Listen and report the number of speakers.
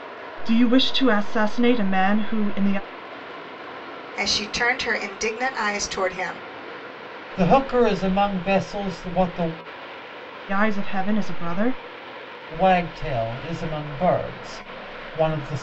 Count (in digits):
3